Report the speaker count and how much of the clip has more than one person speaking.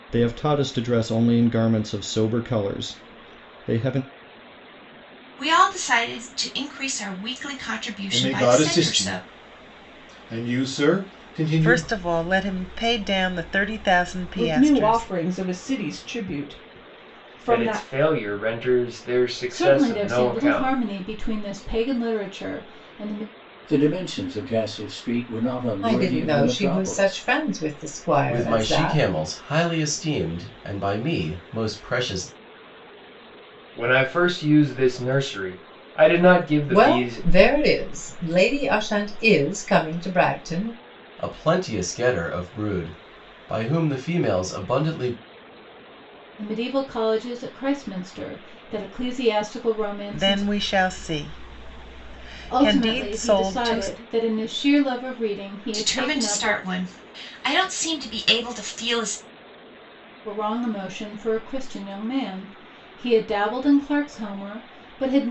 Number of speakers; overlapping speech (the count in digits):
10, about 15%